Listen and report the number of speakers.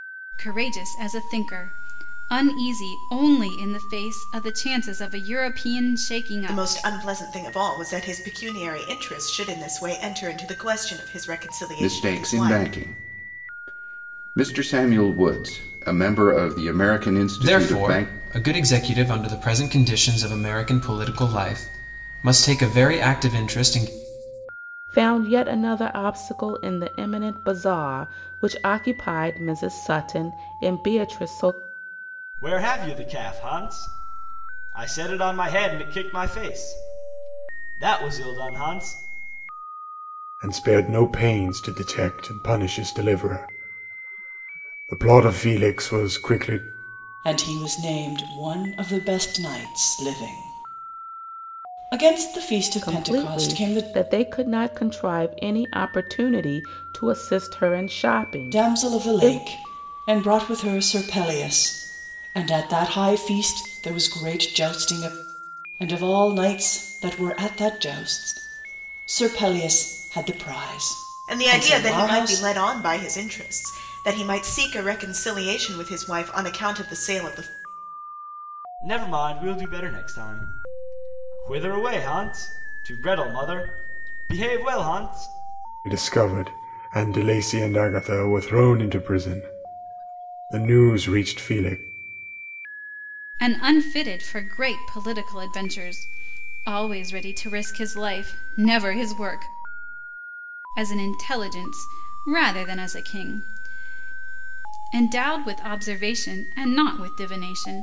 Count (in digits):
8